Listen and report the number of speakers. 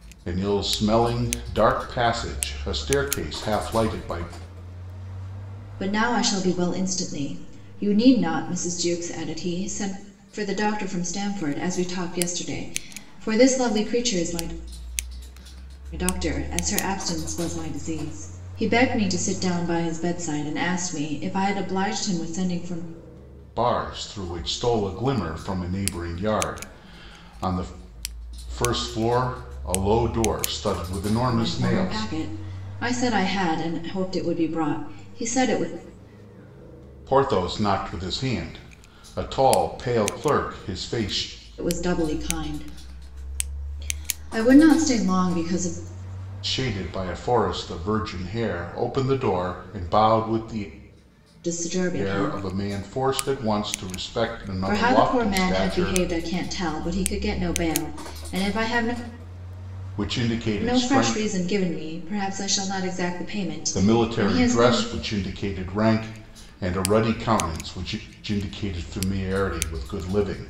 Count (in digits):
2